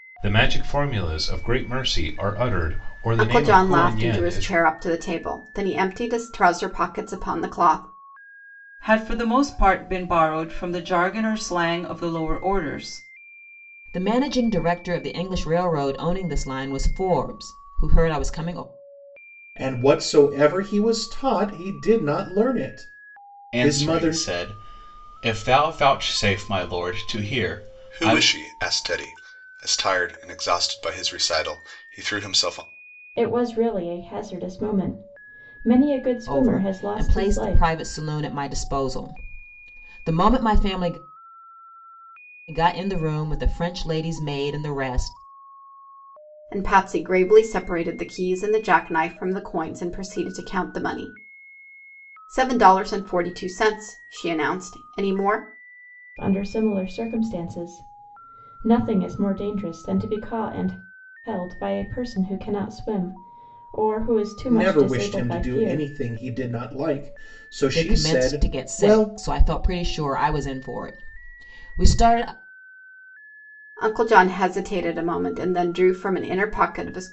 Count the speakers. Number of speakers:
8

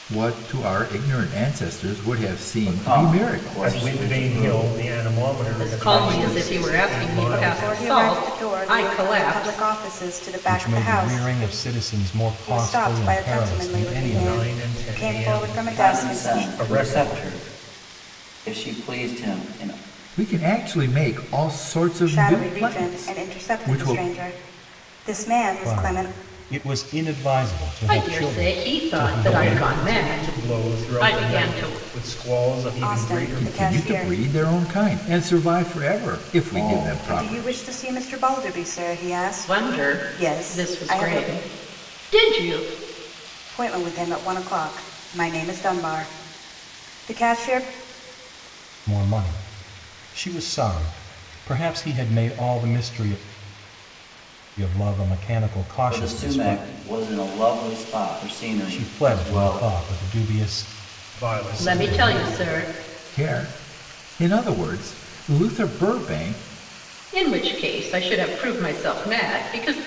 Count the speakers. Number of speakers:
6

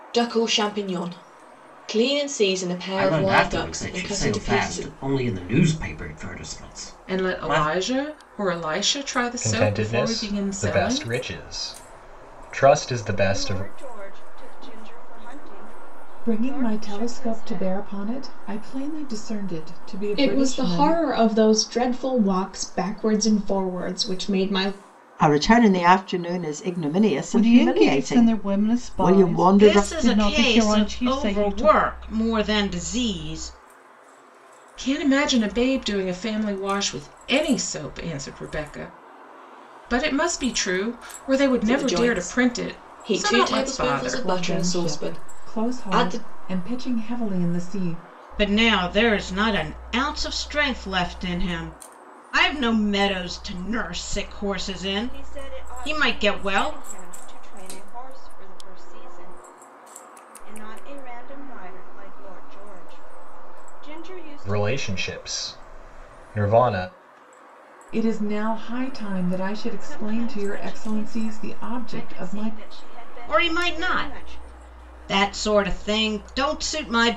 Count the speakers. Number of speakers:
10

